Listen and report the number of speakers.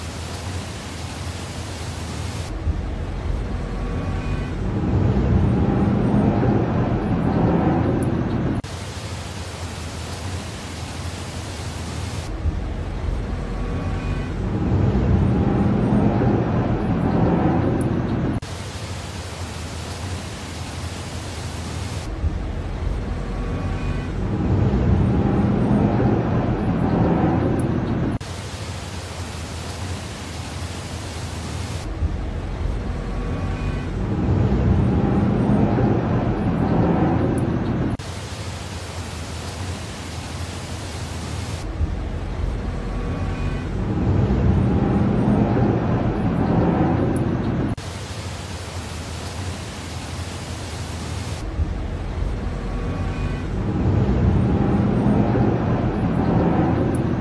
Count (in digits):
0